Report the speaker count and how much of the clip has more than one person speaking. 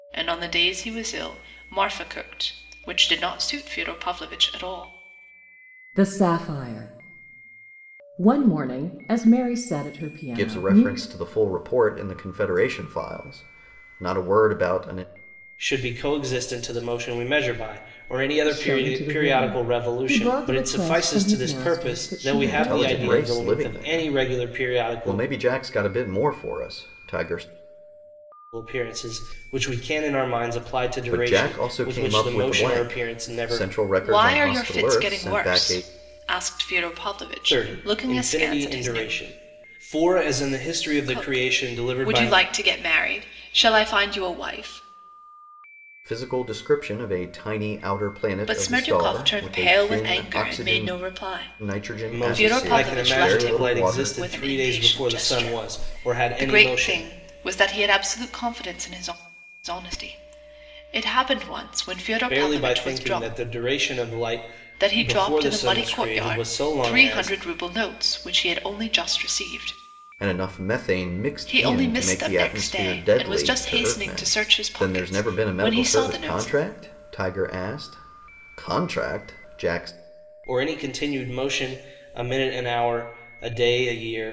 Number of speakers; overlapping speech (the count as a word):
four, about 38%